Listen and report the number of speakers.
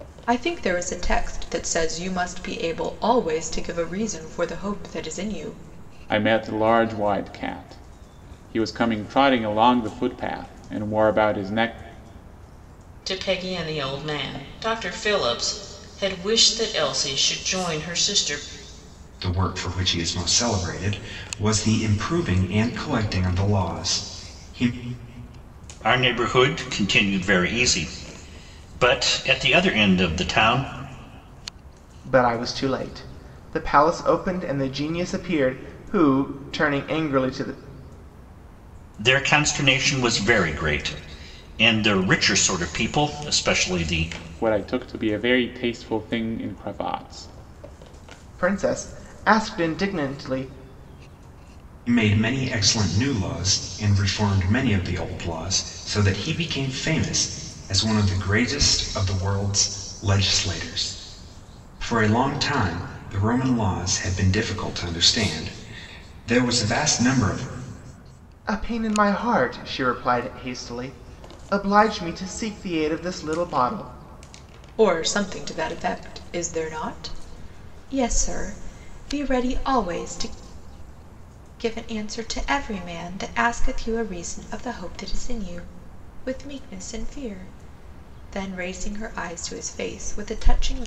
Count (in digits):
6